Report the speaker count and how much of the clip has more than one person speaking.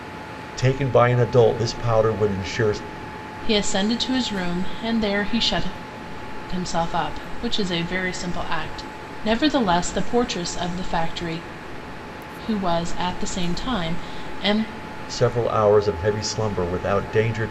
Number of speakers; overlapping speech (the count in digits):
2, no overlap